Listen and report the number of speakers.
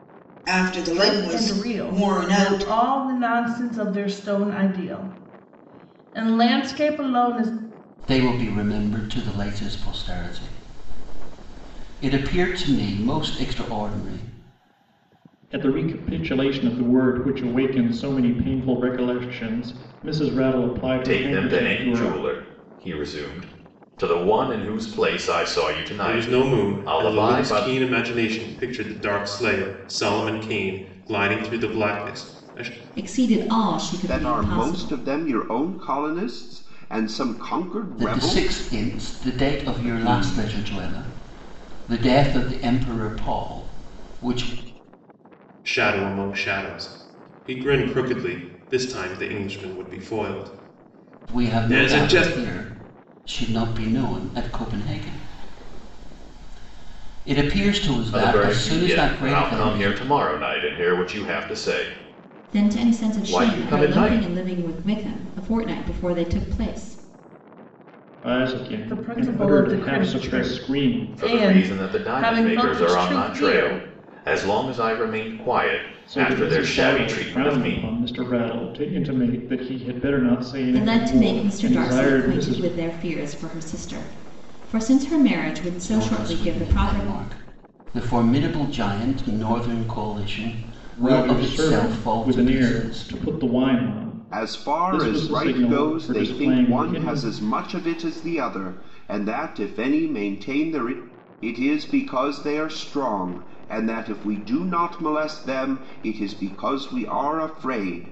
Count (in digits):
8